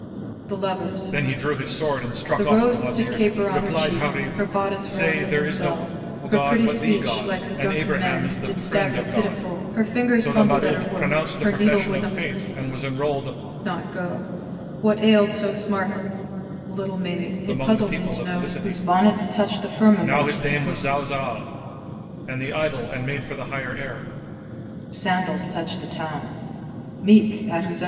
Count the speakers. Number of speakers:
two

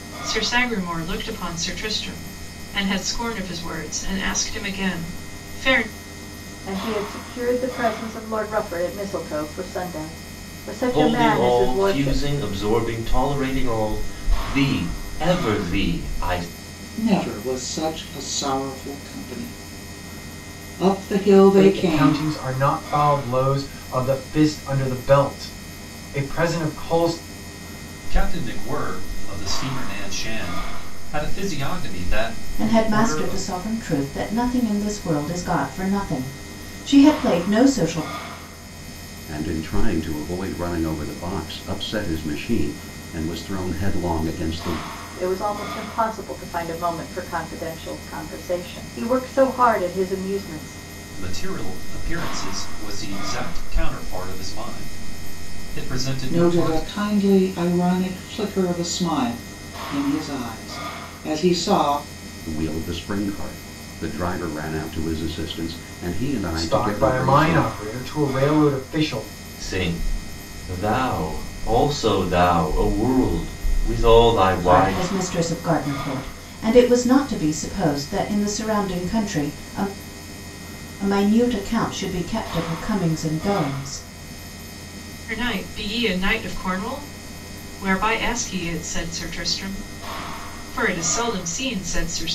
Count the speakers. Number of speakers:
eight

